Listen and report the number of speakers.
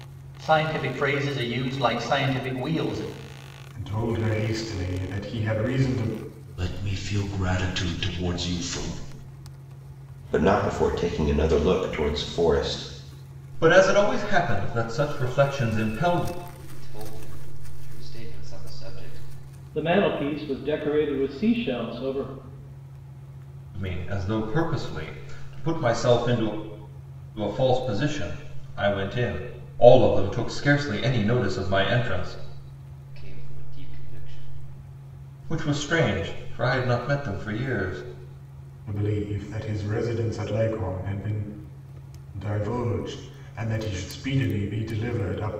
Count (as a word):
seven